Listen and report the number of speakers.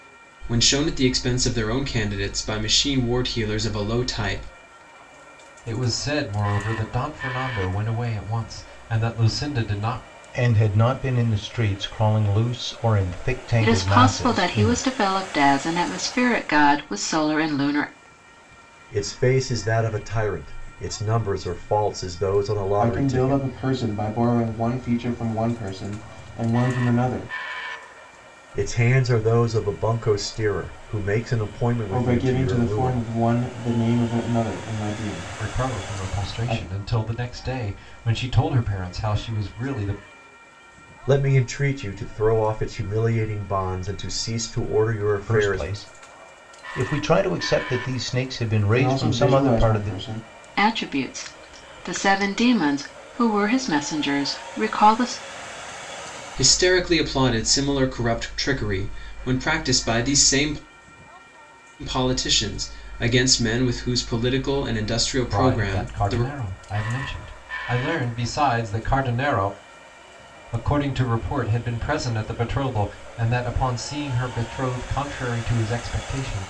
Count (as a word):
six